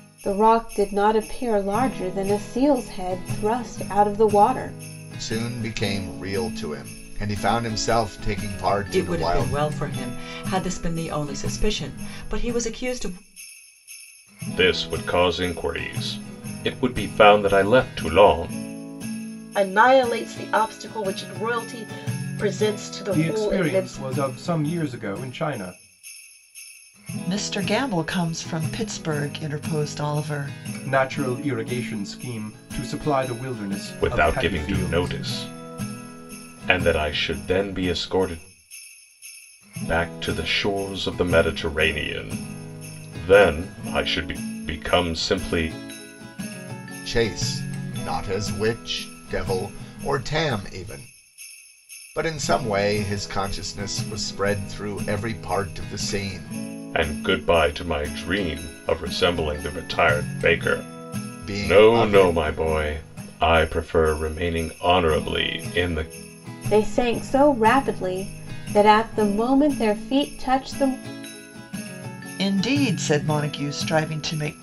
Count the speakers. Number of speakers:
7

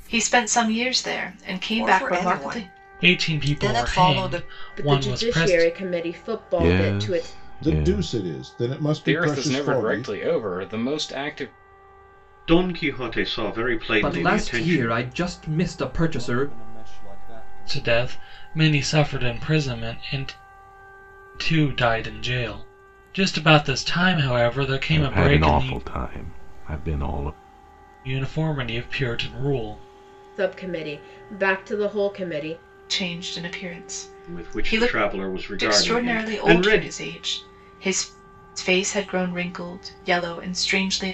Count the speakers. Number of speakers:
10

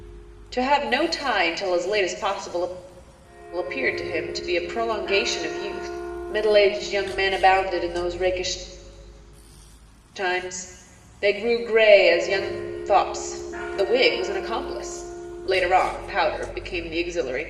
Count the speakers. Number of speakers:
1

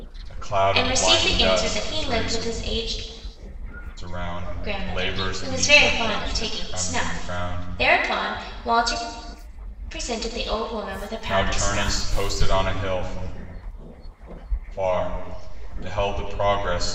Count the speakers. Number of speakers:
2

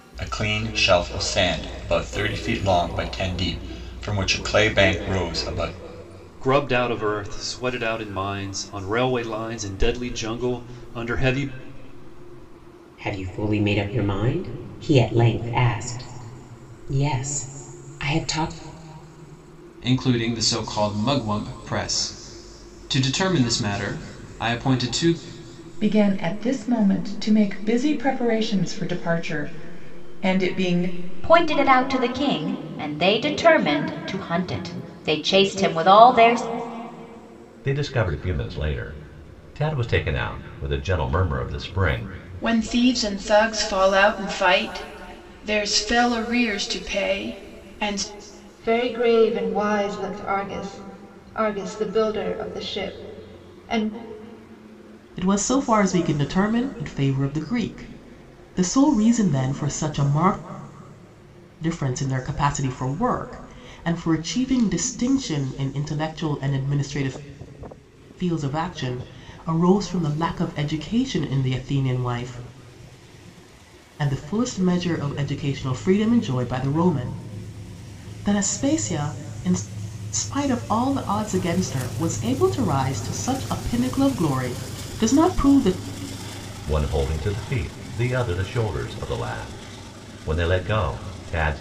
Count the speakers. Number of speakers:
10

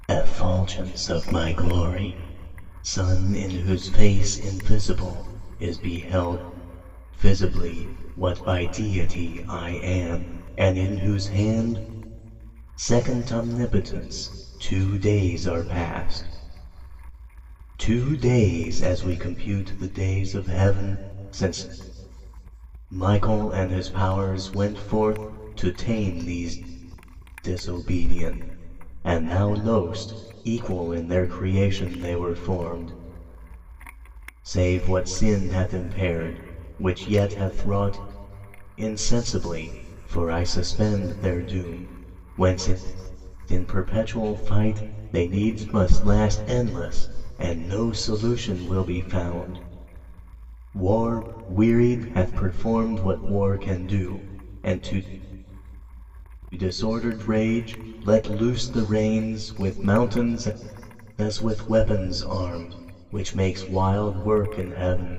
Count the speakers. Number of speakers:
1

